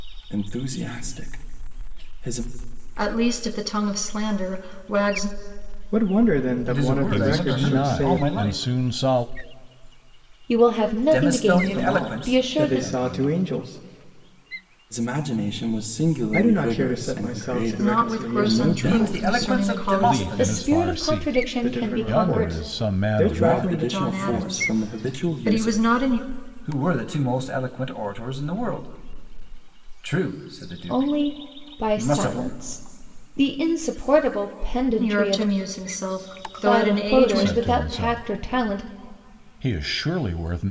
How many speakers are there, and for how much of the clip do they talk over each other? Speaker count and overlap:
6, about 45%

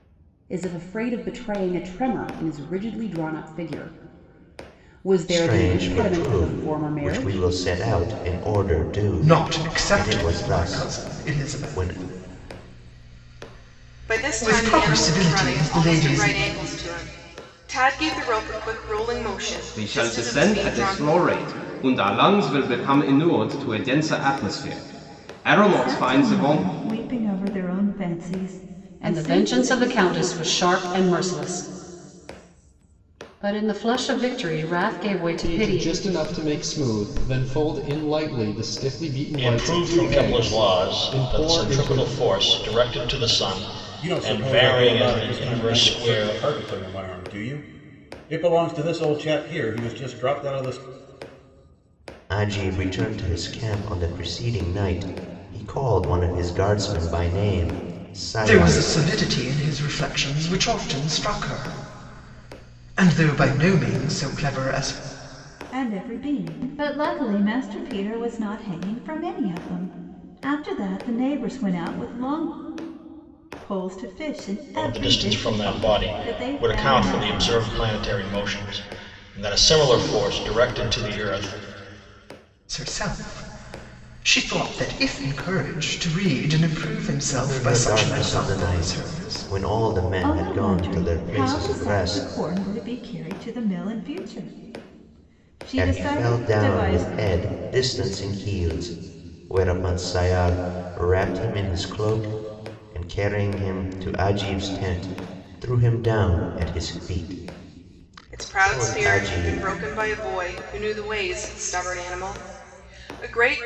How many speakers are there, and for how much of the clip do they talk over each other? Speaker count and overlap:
10, about 24%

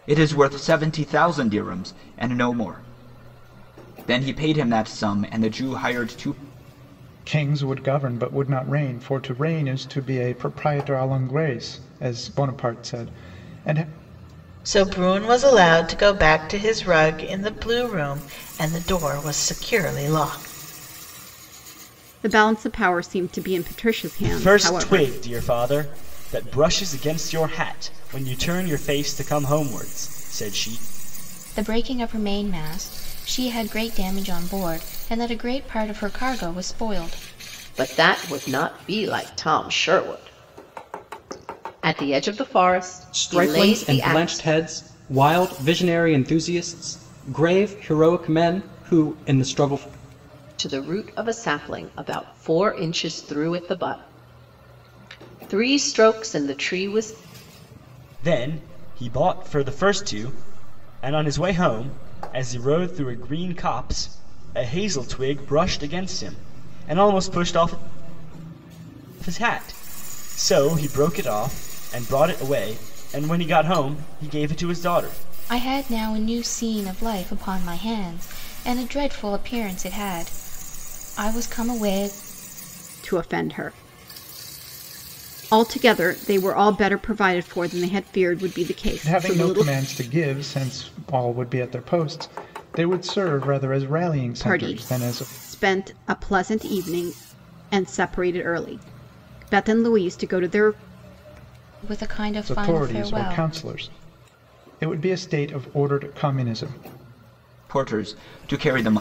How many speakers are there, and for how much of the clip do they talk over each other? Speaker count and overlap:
8, about 5%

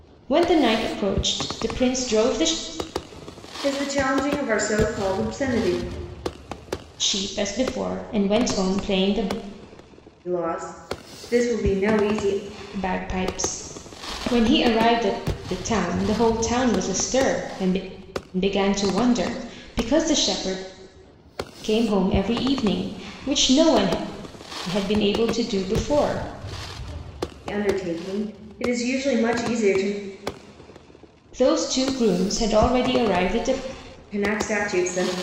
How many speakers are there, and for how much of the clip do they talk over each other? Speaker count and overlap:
2, no overlap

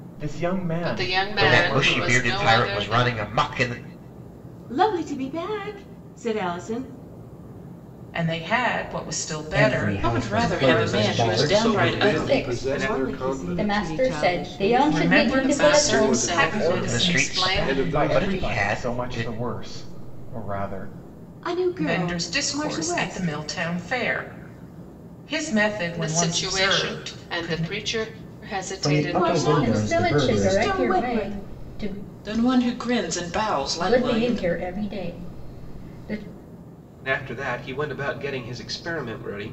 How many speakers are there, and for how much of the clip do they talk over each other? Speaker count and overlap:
10, about 47%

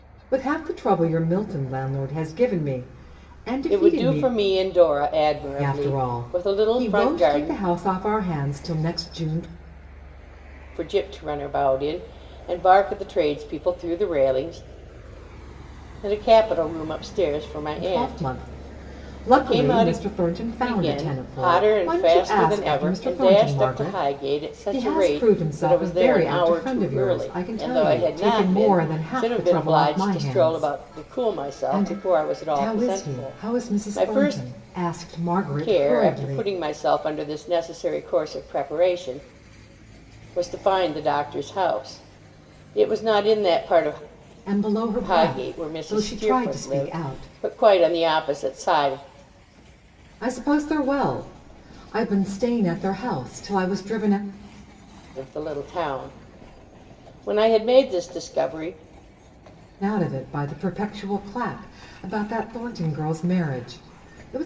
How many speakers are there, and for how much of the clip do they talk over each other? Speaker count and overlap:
2, about 32%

